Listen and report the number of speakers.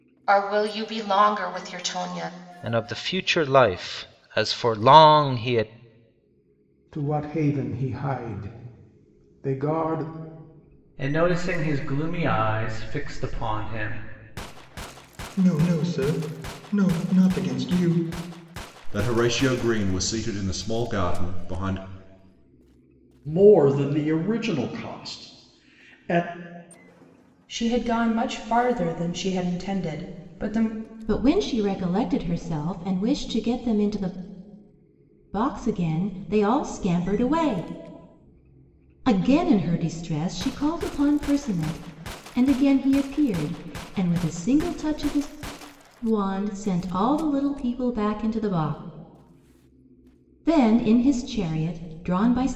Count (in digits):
9